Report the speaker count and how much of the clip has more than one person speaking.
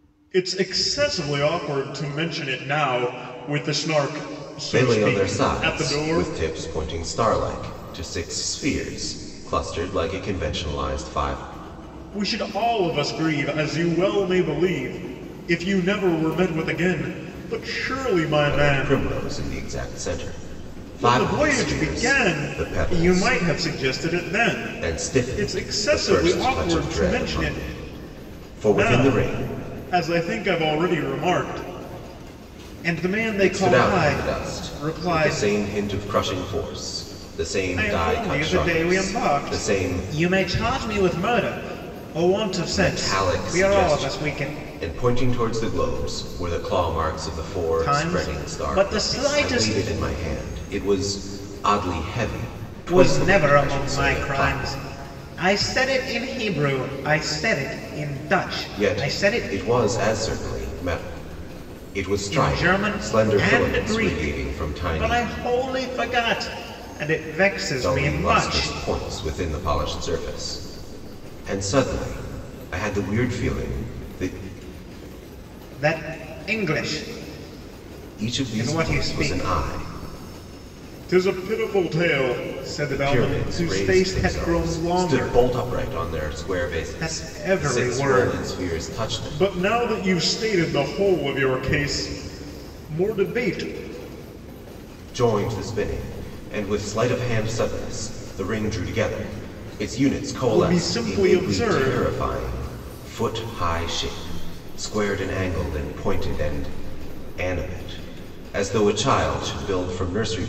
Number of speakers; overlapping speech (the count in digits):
2, about 28%